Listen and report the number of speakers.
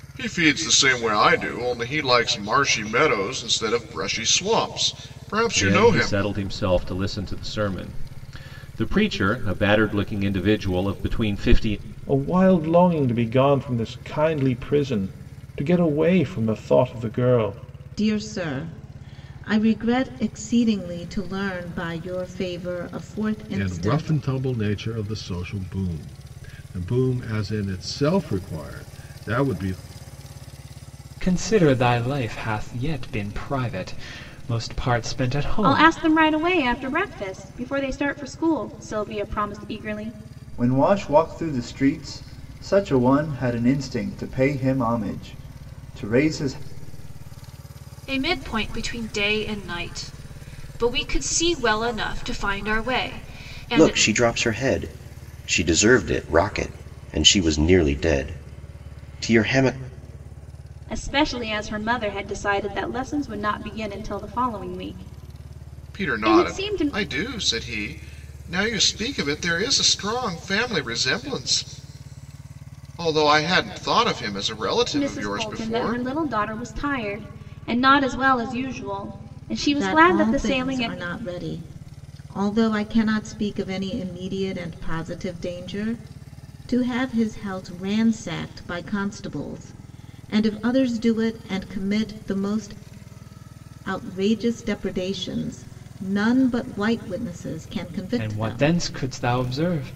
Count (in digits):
10